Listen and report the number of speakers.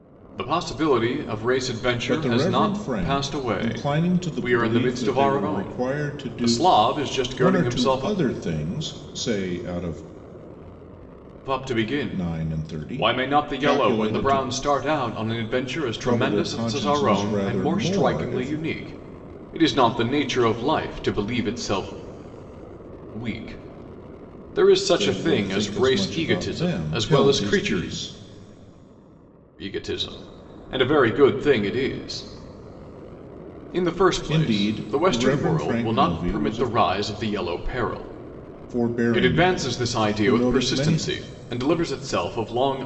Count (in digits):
2